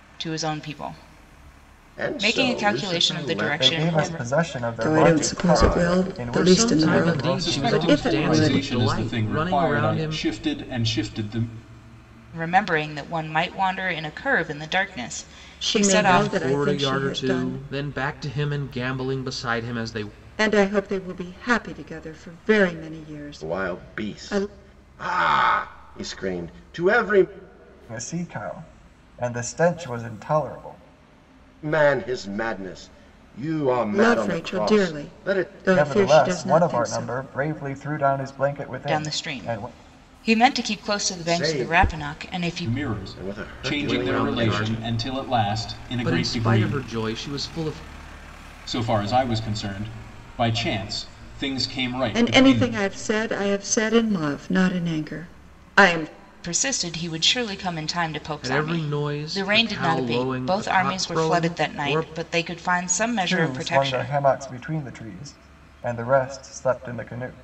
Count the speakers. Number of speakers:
6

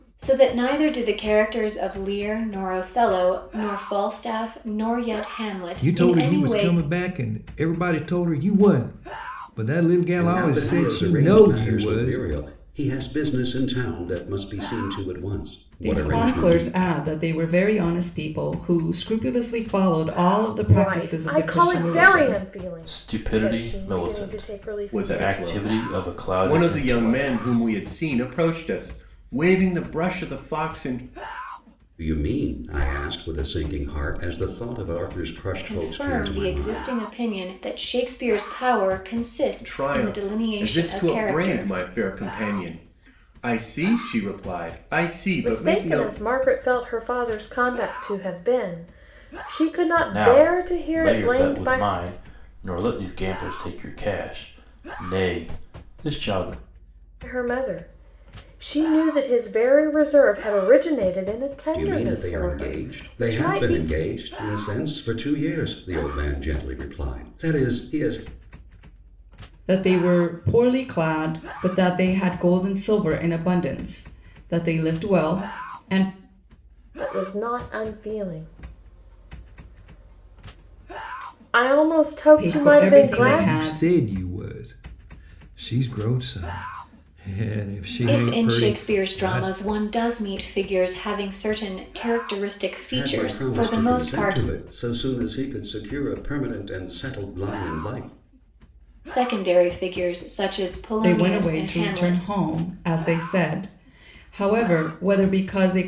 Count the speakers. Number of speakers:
7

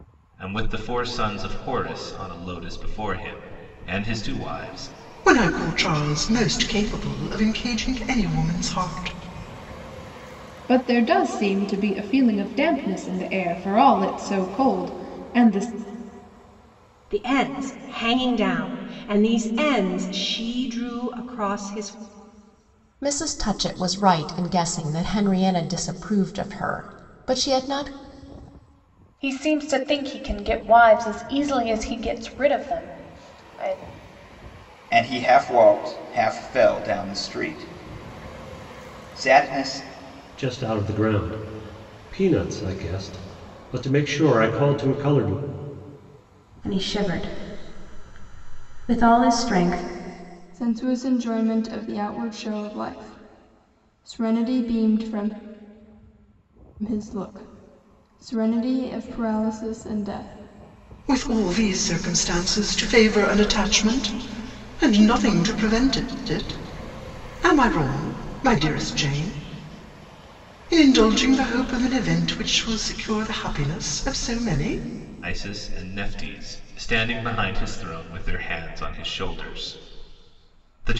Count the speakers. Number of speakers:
10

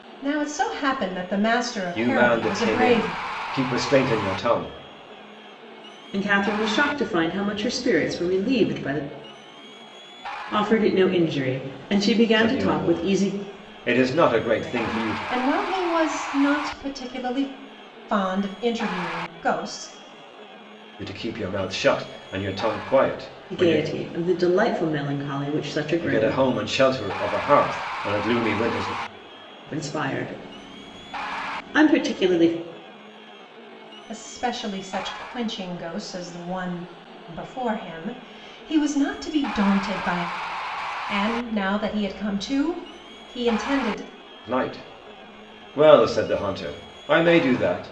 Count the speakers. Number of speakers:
3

